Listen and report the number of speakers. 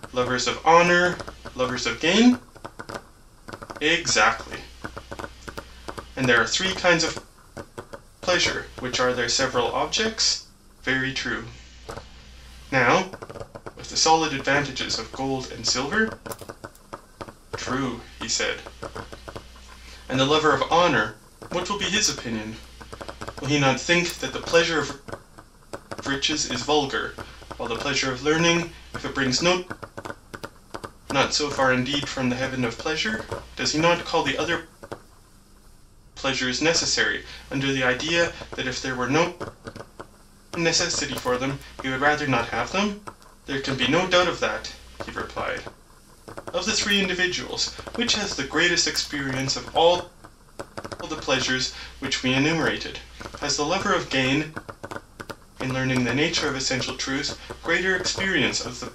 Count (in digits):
1